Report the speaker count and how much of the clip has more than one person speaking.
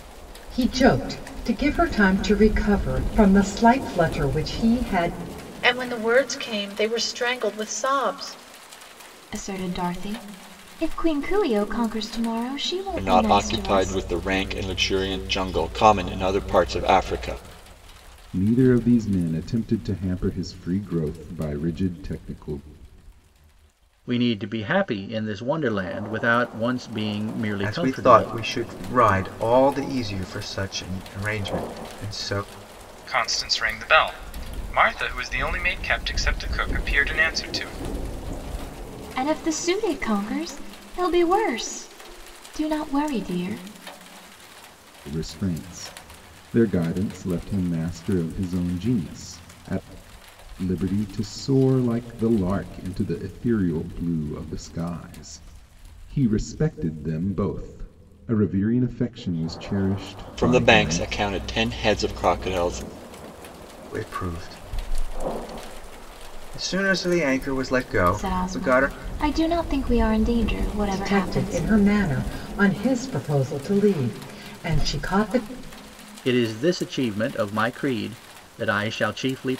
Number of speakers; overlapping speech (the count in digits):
8, about 5%